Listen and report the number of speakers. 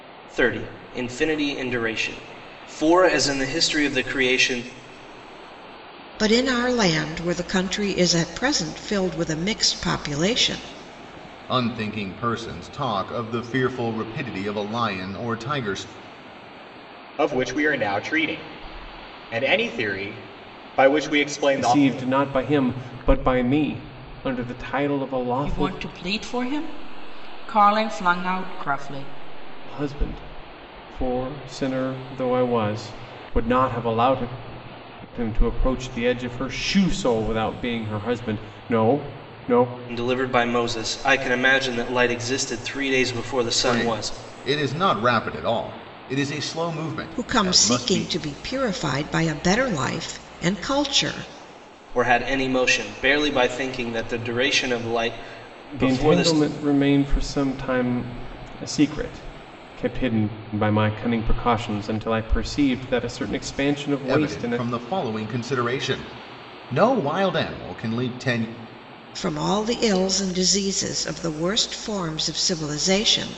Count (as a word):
six